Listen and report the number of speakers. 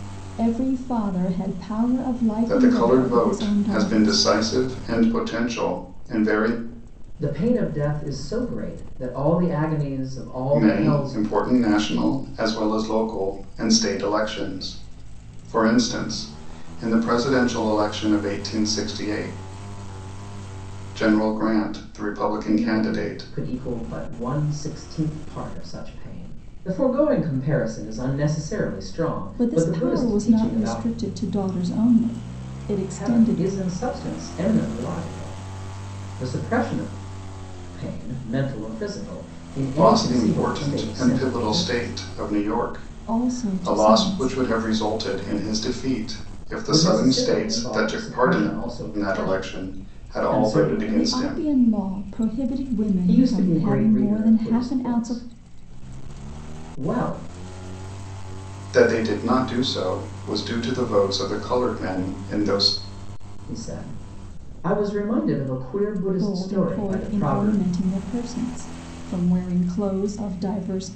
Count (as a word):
three